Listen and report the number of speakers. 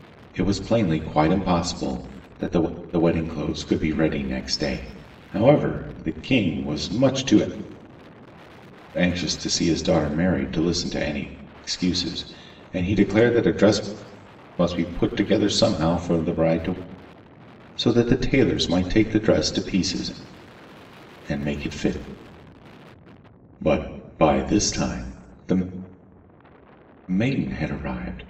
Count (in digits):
1